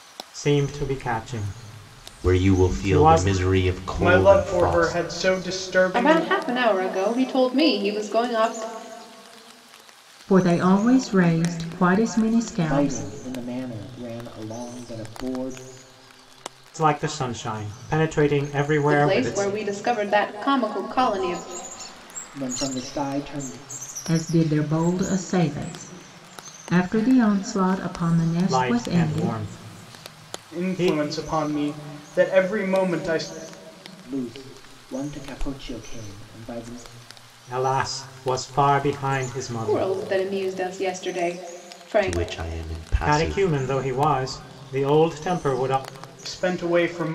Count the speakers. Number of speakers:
6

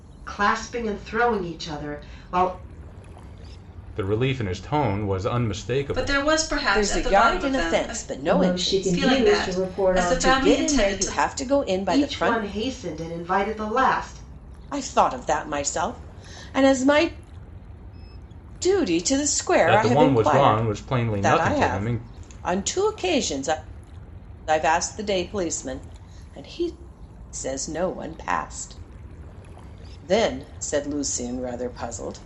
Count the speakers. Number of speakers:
5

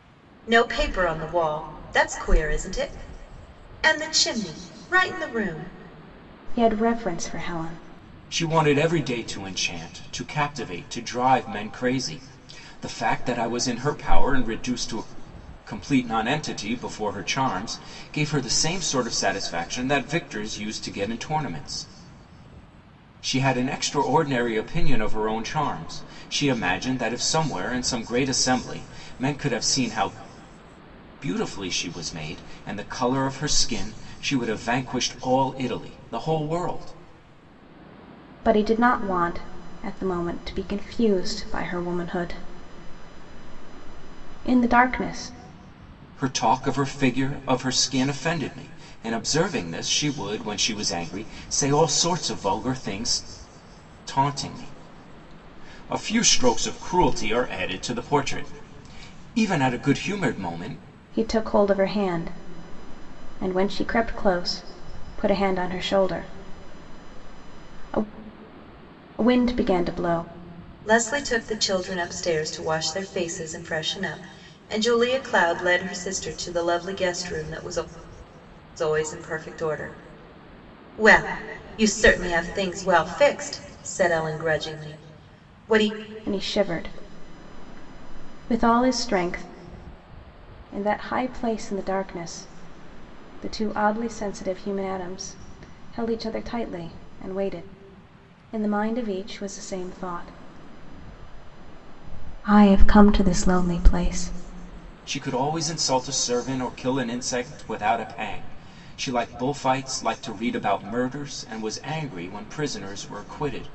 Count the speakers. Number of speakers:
3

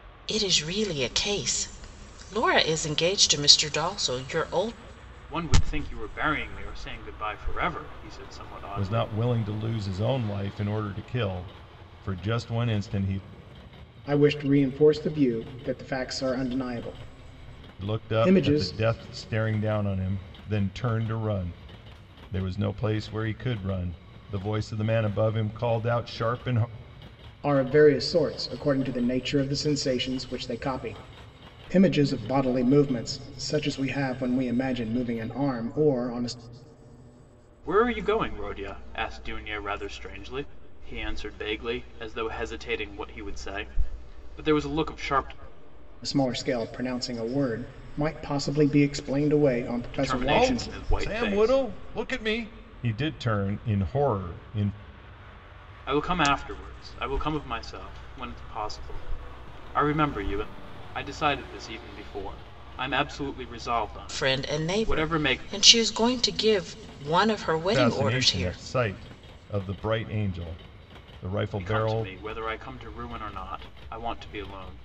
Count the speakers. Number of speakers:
4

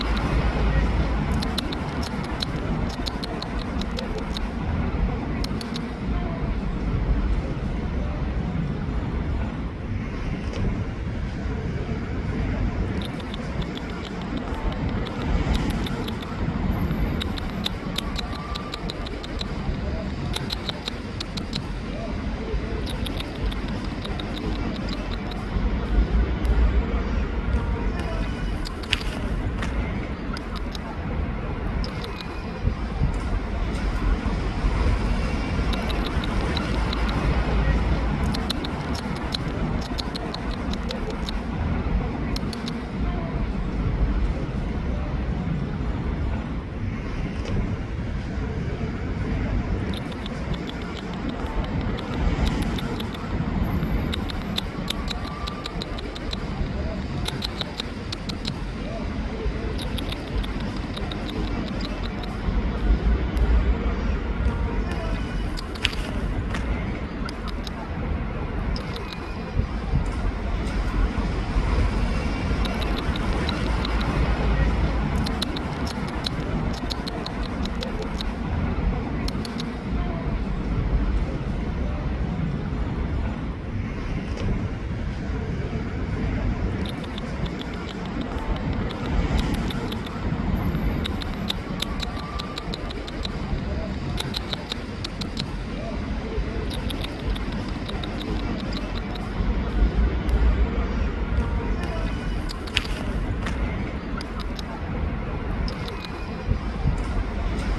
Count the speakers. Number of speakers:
0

